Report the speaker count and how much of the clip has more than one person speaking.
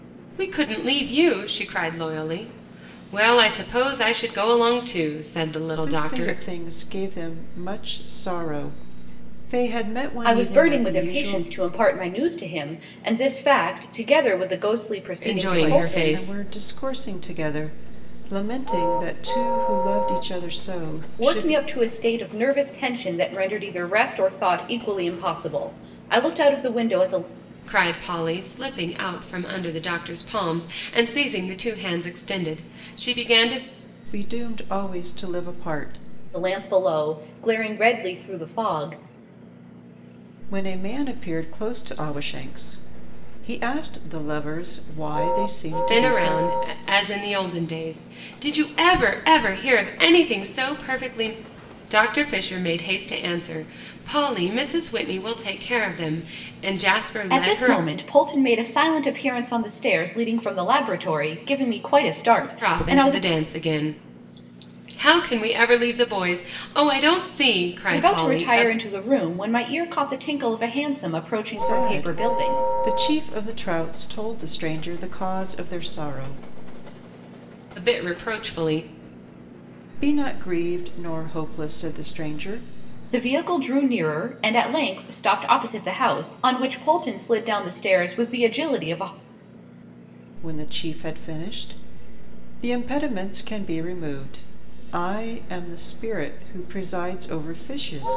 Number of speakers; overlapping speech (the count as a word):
three, about 7%